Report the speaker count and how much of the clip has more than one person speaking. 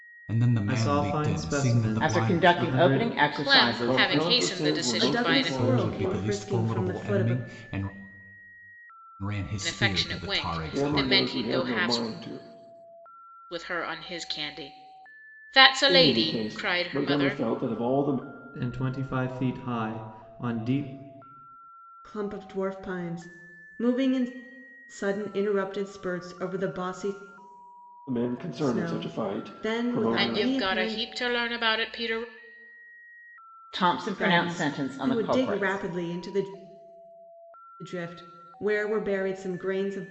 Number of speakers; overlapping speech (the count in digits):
6, about 37%